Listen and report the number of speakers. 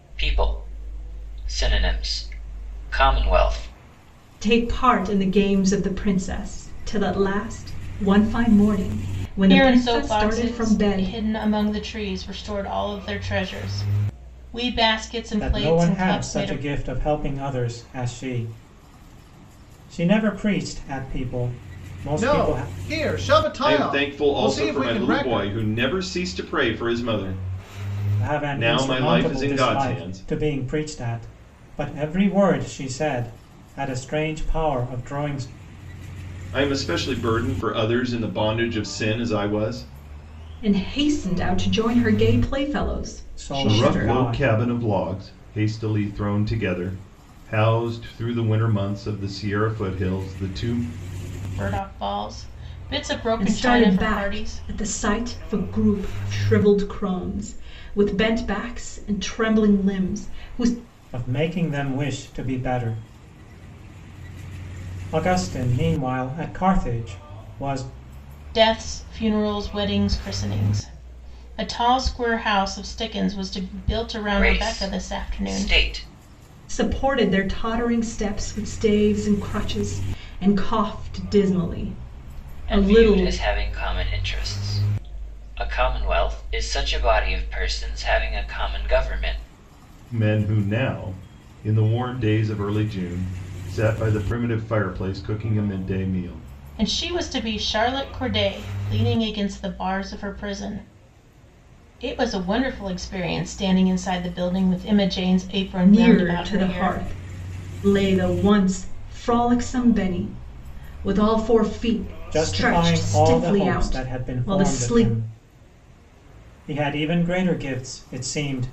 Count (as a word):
six